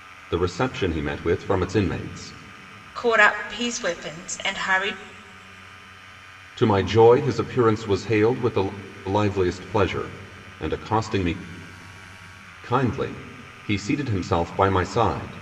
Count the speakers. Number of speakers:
2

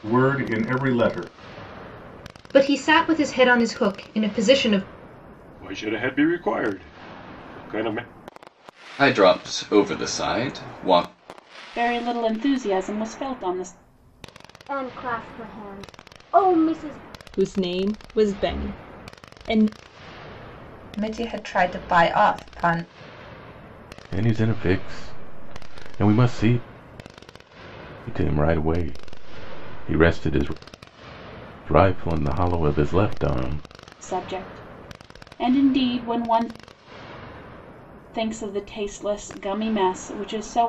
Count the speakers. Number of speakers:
9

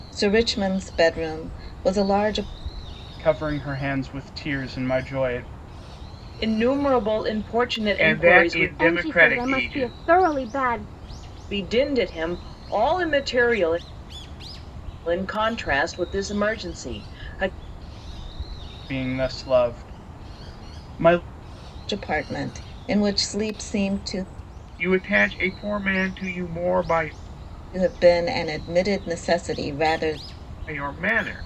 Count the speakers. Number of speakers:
5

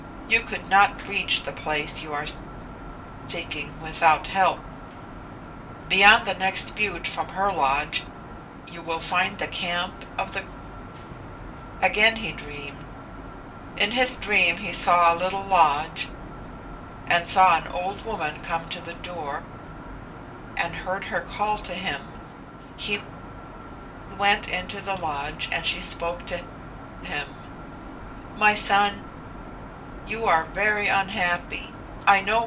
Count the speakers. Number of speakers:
1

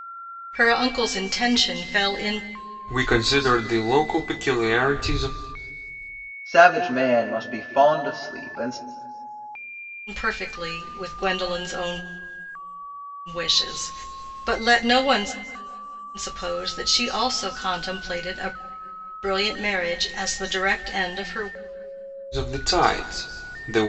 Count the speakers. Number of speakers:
3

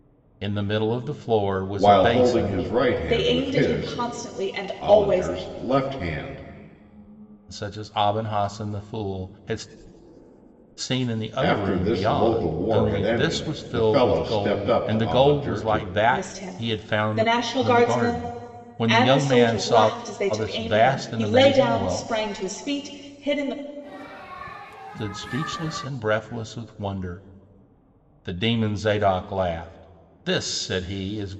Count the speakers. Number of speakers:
3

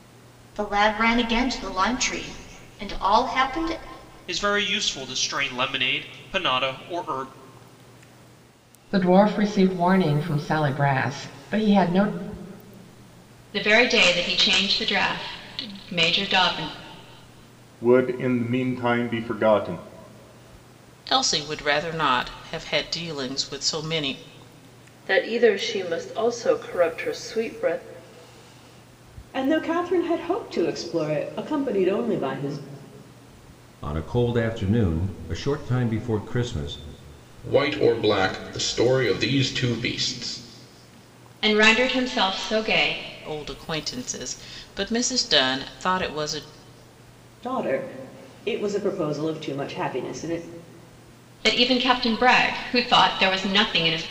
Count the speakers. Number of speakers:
10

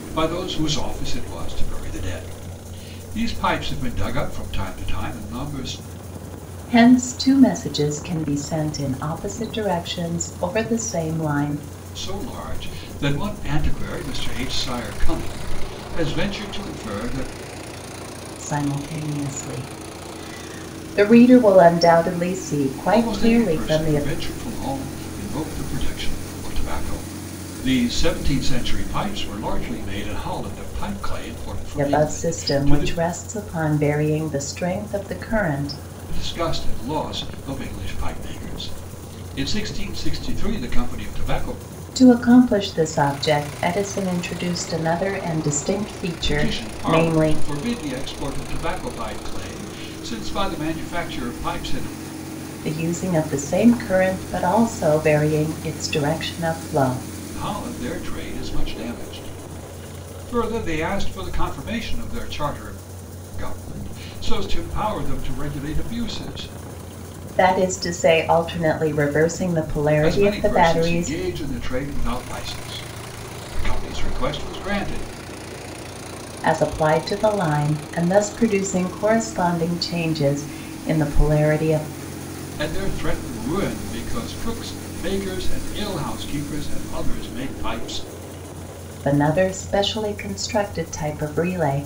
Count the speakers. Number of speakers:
2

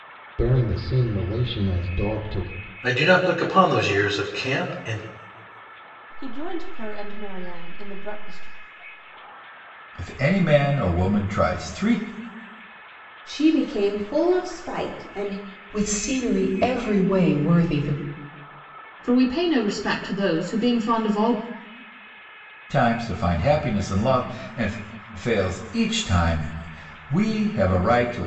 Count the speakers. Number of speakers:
7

